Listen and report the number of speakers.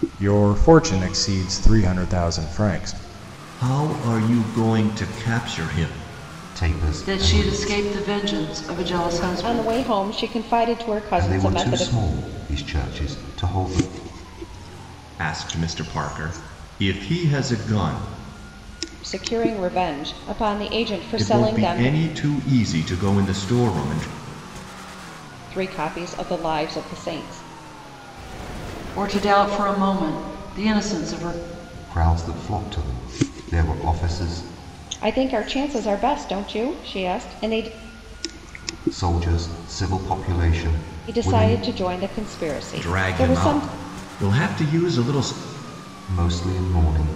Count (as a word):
five